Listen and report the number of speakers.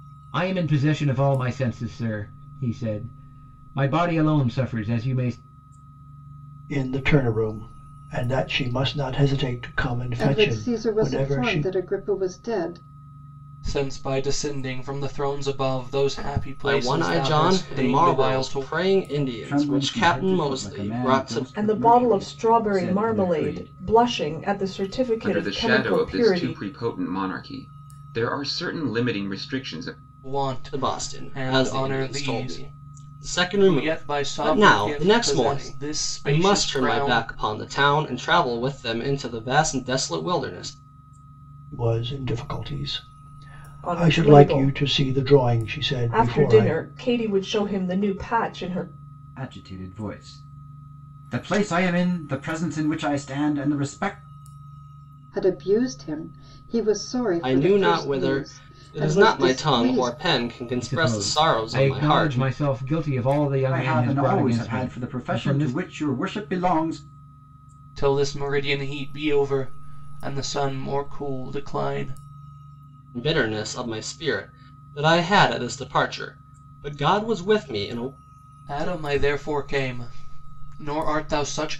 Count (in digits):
8